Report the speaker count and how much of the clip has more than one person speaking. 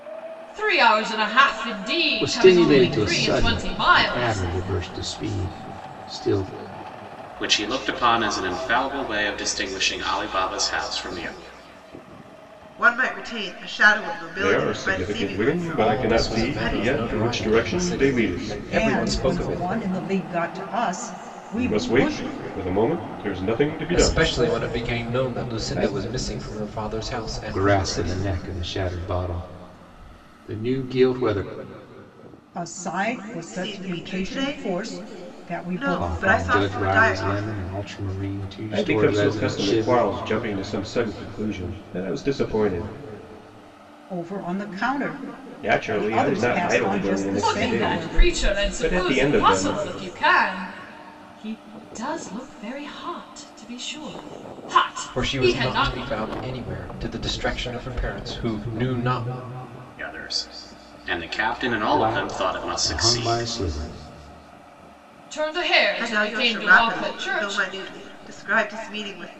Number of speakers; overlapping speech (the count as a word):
seven, about 36%